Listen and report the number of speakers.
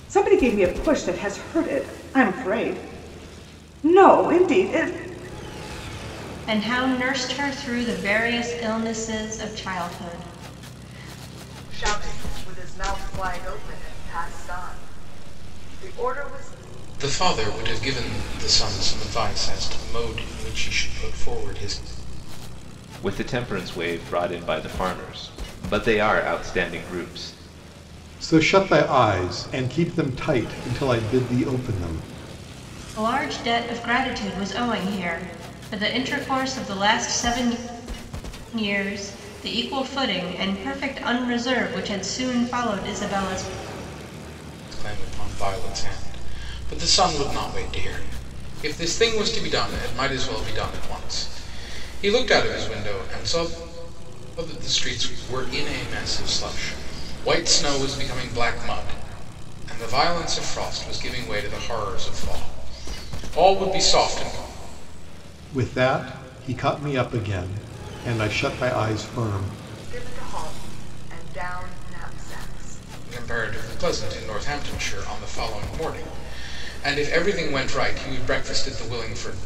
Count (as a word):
six